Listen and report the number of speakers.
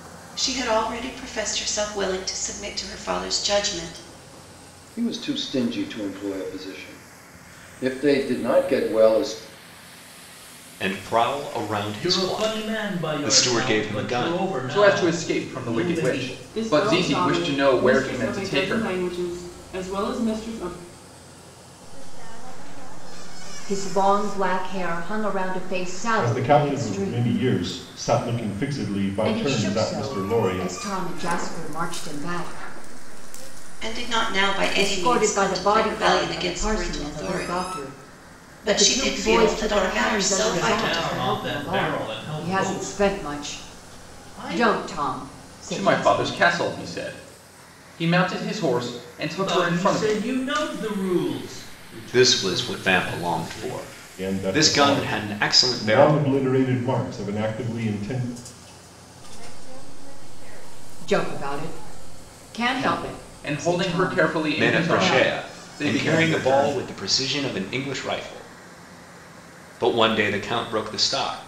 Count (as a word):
nine